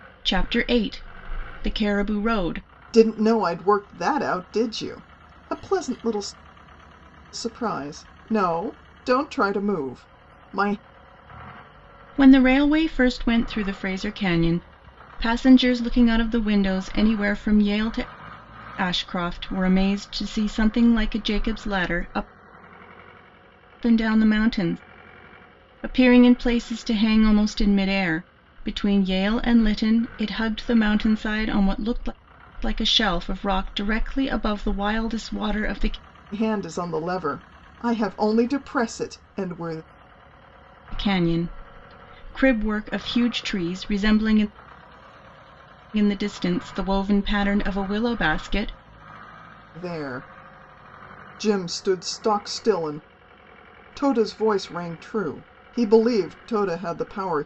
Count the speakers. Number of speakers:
2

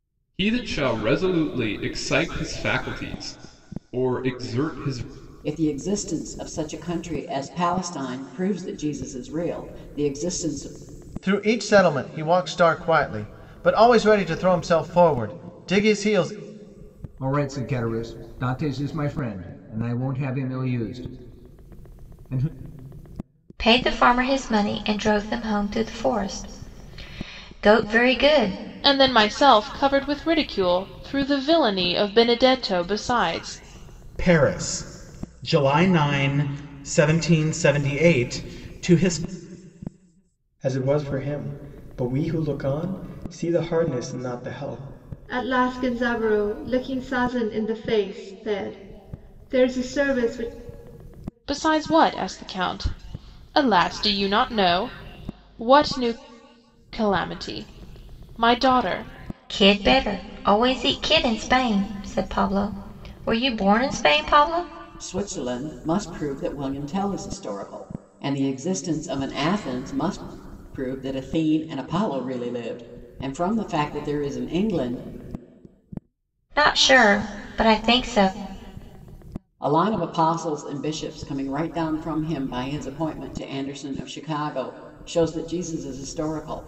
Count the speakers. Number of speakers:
9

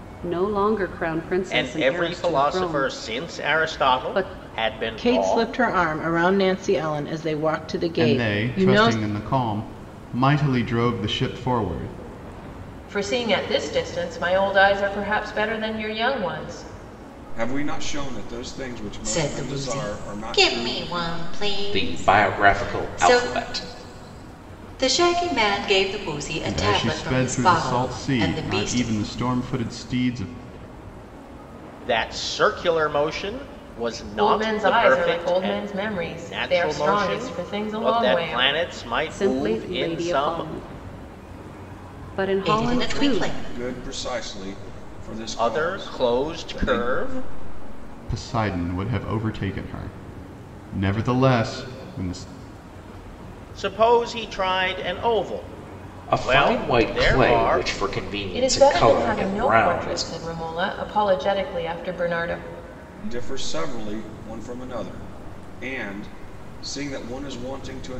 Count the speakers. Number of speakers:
8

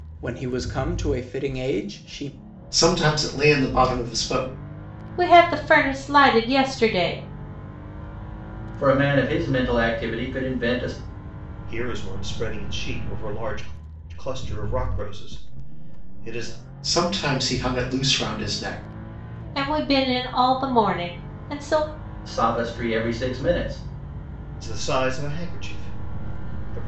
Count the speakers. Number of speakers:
5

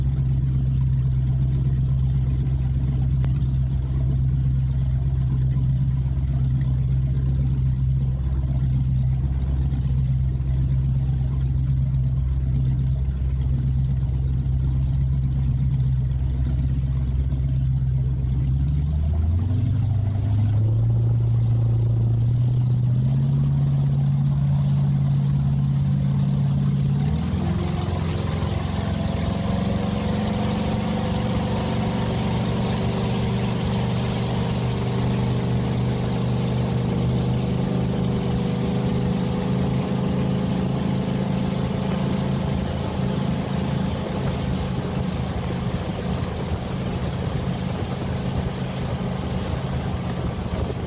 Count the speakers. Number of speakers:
0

